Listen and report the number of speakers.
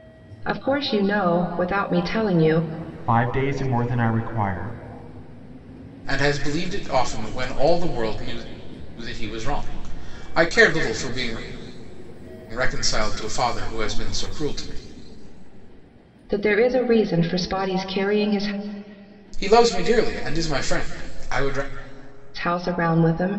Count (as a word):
three